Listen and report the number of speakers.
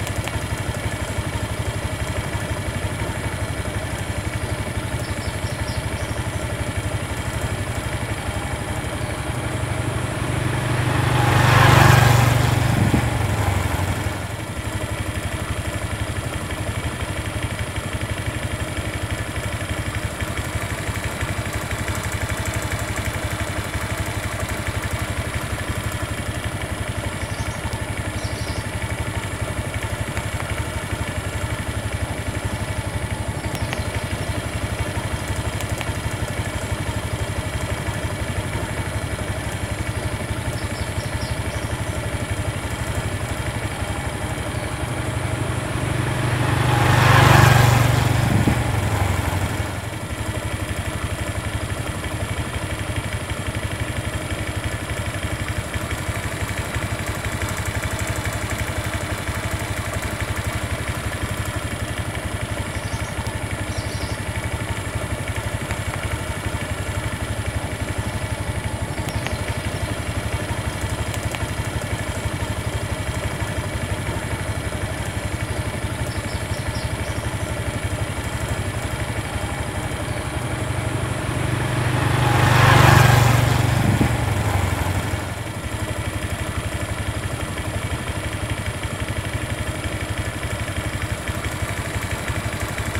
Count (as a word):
zero